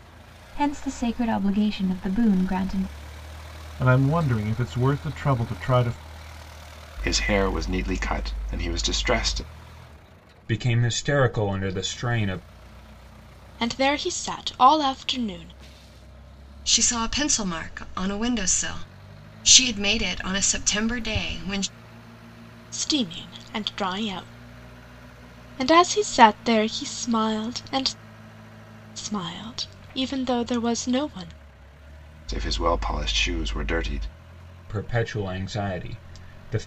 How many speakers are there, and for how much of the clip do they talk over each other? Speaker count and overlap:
6, no overlap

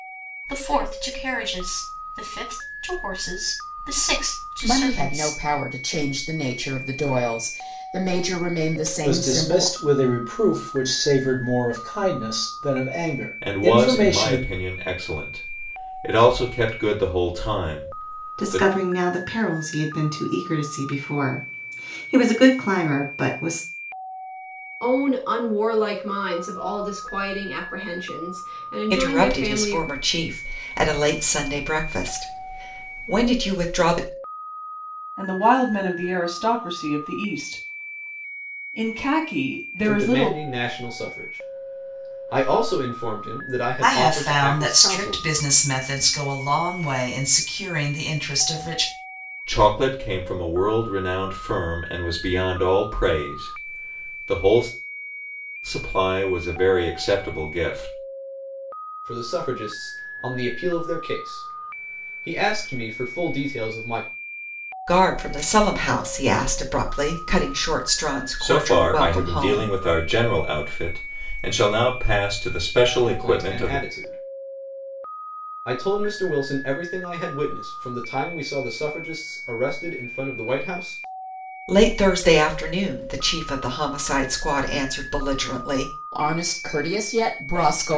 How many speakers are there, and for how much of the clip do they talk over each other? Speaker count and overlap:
10, about 9%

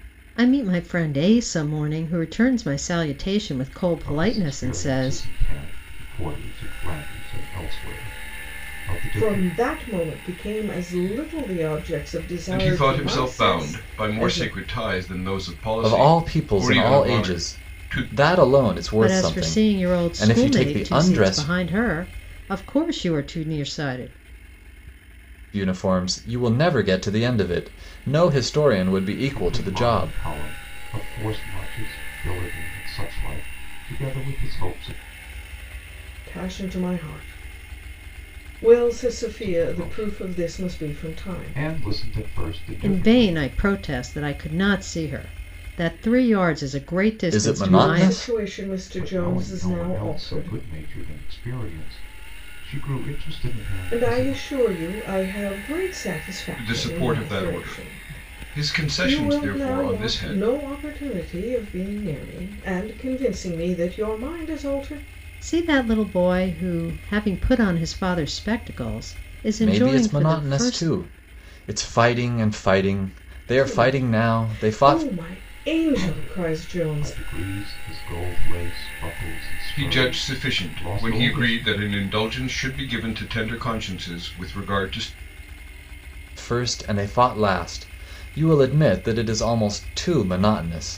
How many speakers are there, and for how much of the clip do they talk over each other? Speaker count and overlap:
5, about 28%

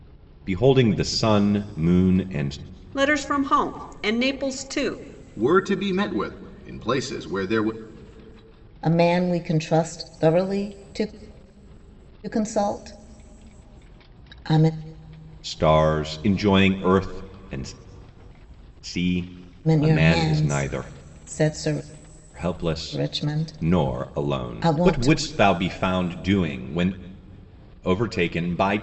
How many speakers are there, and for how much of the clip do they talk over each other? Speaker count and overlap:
4, about 12%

